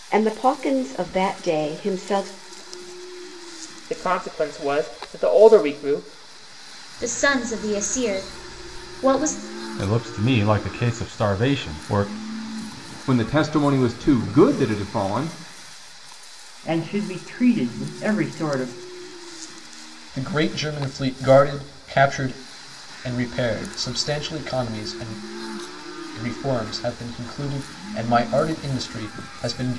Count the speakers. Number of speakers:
7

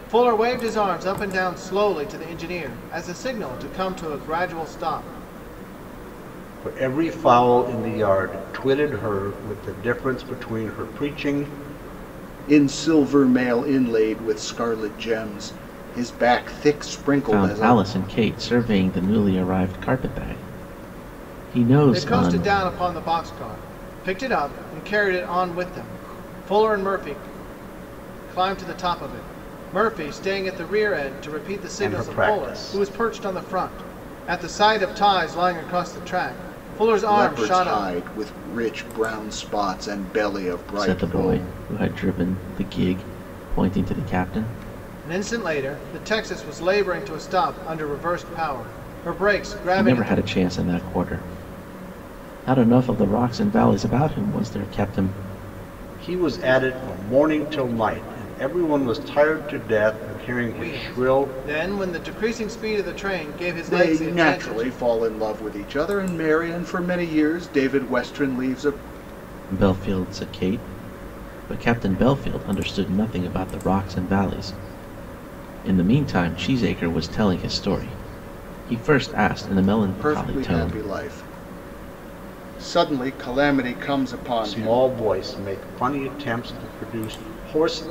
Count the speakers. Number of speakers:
4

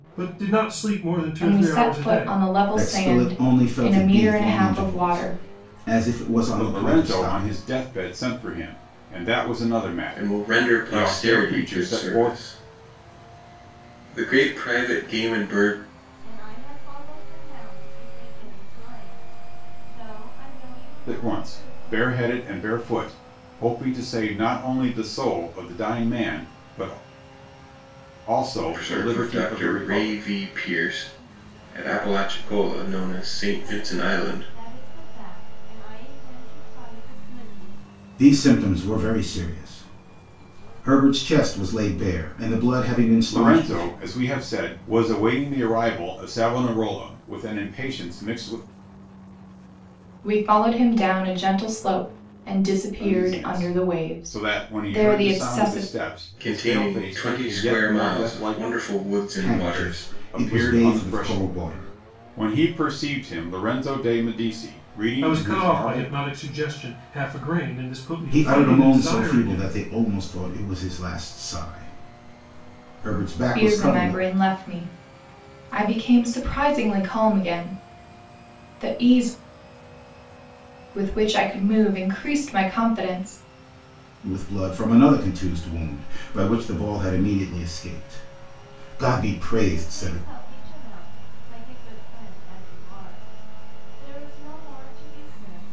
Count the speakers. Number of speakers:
6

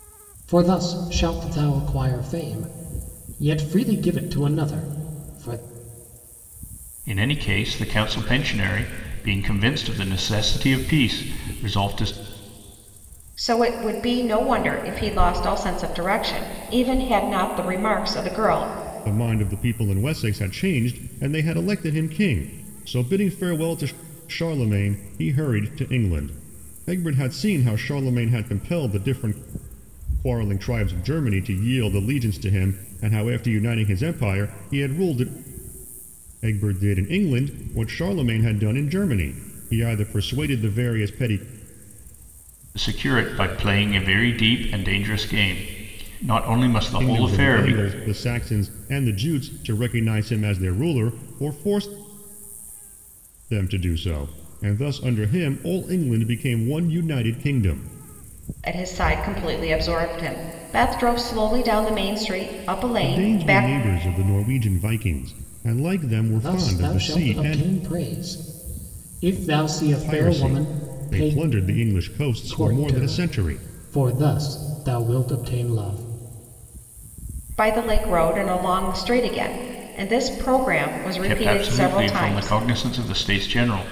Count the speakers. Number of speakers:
4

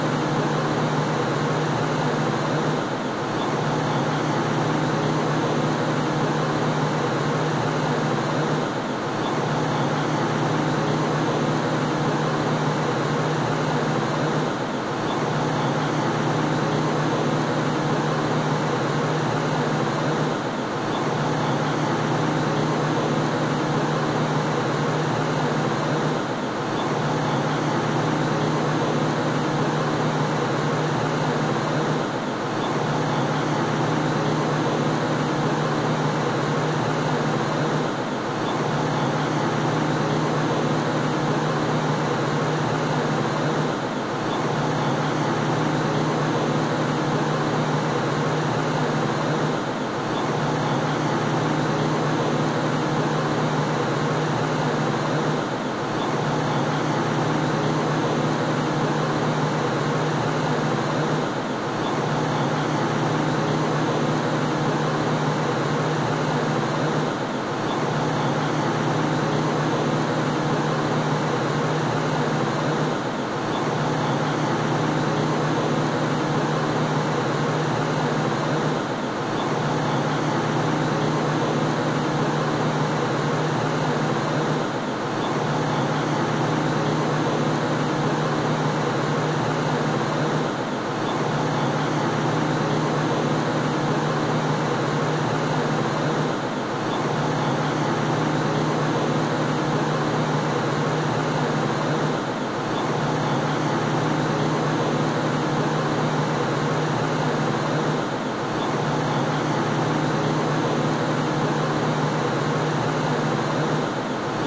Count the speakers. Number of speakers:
0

